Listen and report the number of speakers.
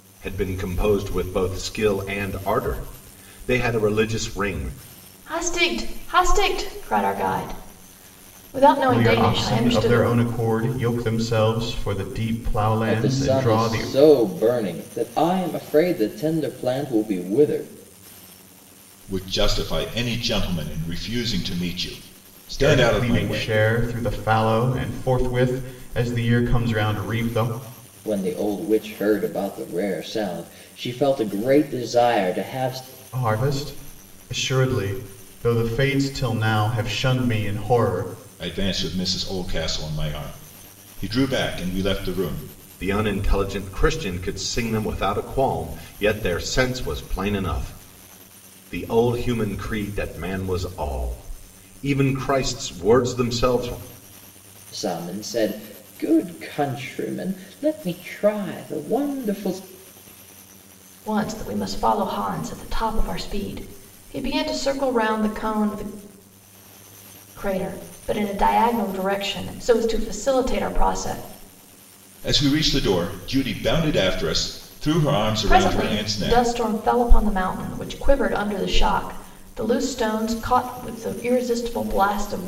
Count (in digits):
5